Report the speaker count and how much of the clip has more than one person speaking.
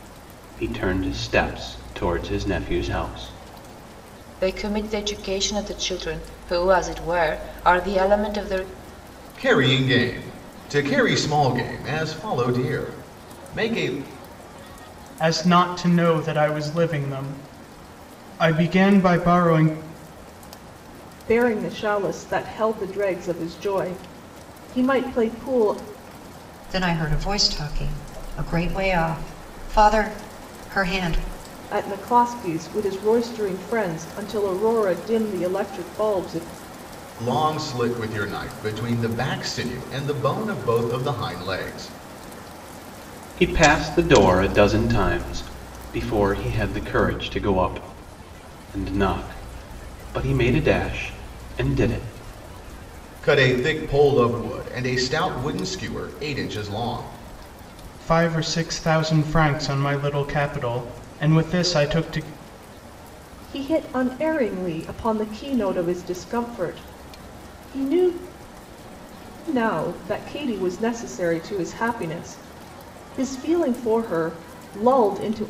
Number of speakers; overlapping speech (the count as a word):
six, no overlap